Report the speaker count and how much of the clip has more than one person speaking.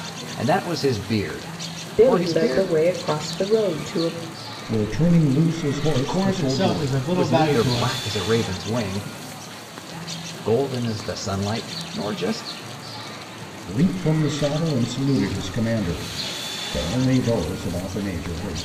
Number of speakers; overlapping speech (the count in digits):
4, about 15%